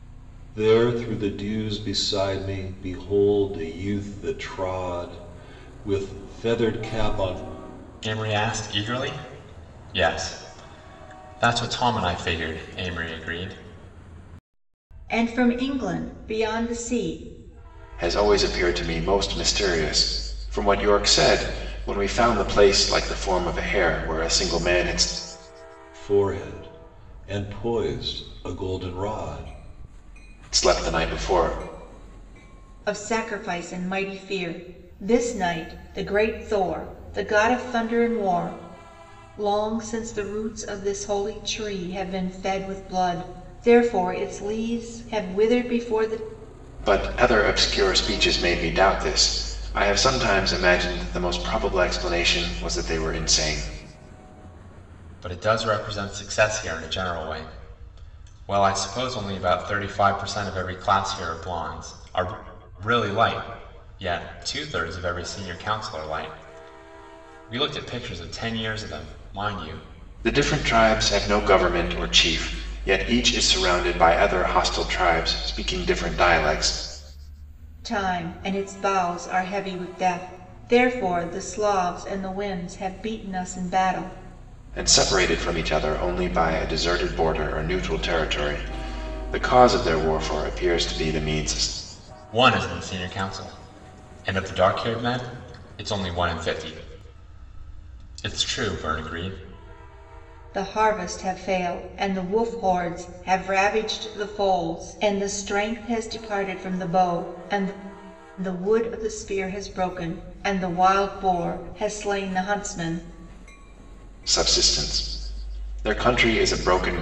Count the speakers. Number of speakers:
4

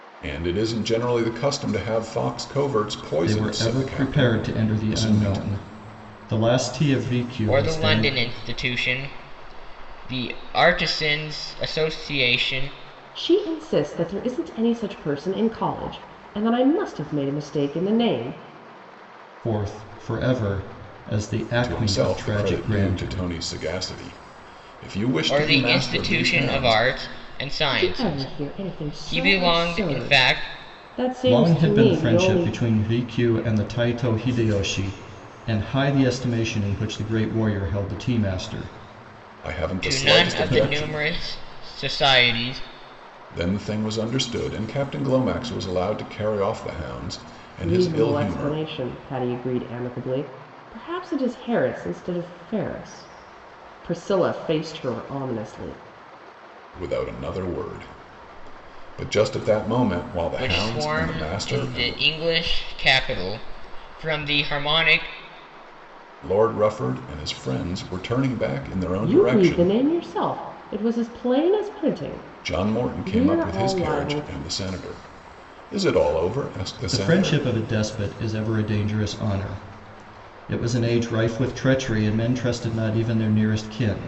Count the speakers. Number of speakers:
4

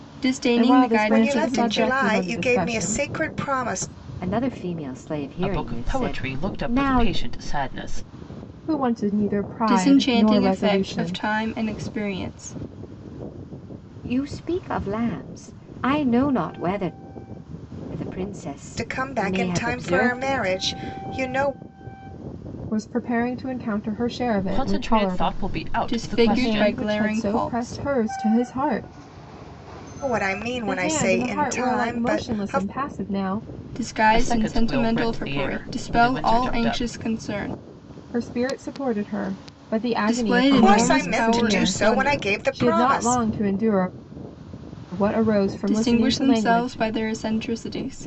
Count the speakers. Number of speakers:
5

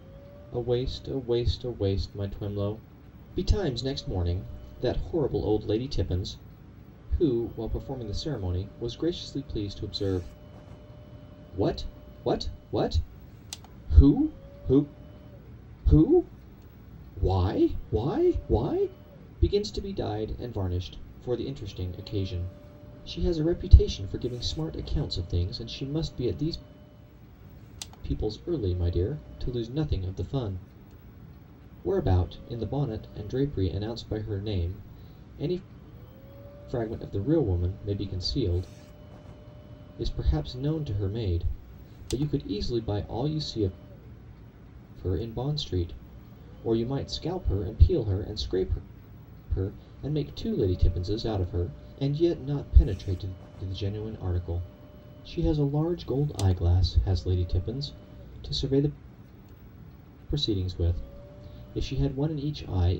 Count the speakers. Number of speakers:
1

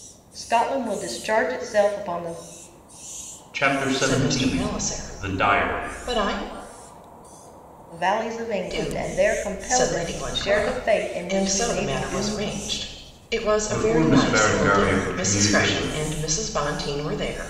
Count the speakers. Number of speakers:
3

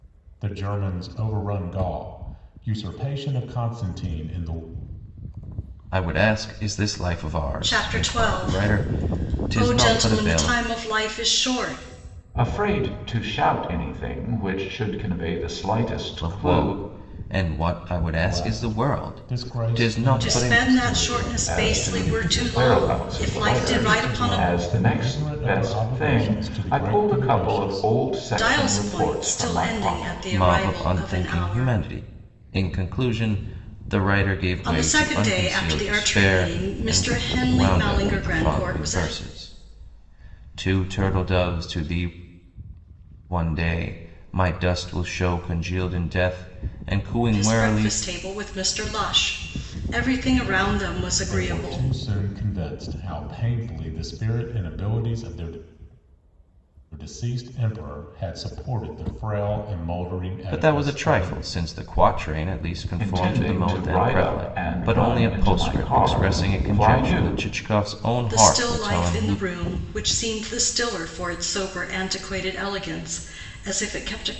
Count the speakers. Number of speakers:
4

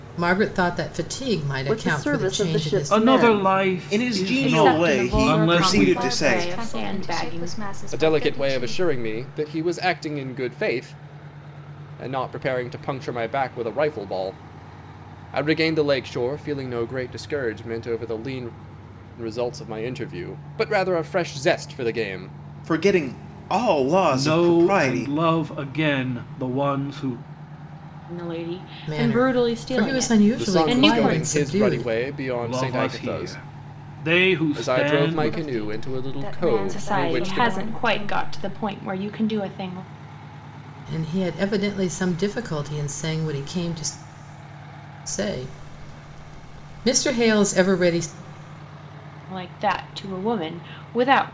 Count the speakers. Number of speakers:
7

